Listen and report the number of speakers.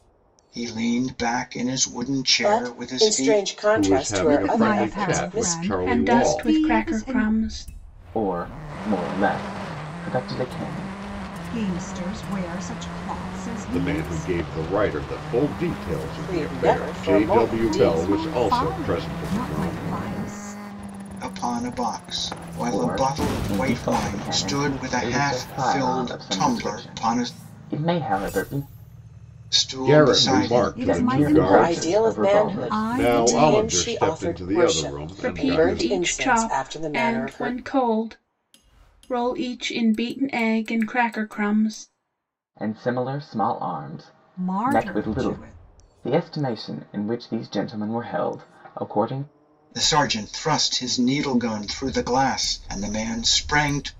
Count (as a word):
six